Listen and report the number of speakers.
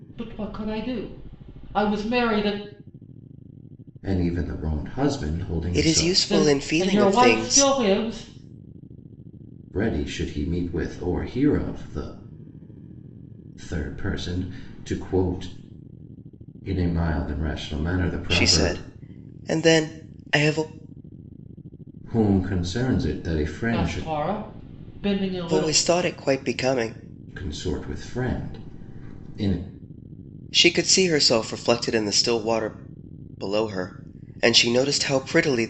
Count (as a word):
three